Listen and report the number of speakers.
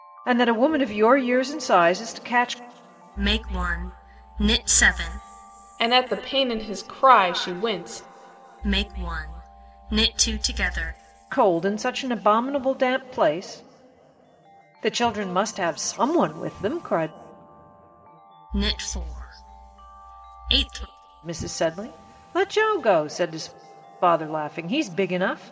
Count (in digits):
3